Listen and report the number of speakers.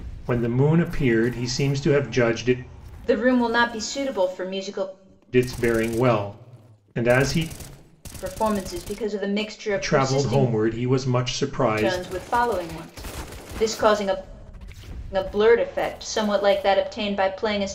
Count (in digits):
2